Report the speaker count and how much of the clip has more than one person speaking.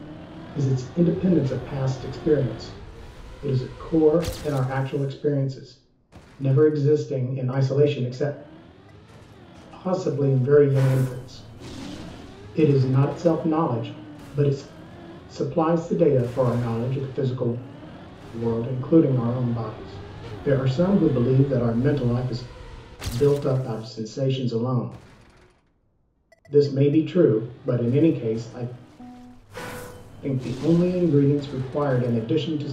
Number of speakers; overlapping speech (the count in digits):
1, no overlap